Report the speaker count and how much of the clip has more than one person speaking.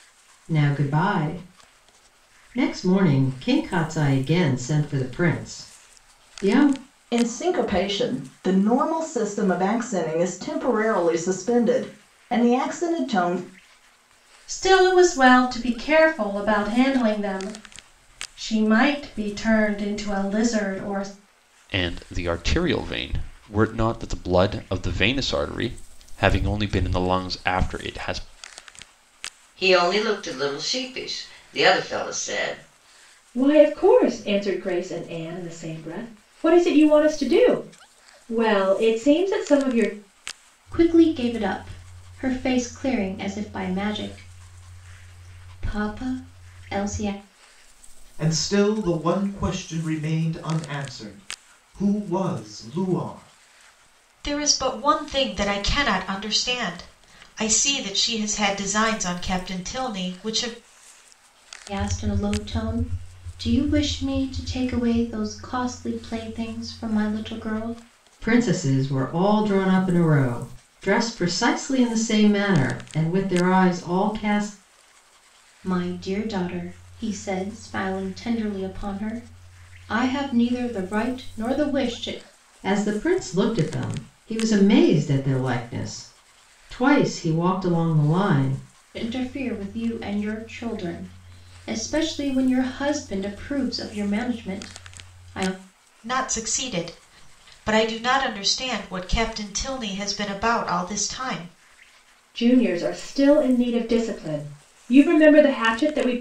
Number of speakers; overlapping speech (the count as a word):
nine, no overlap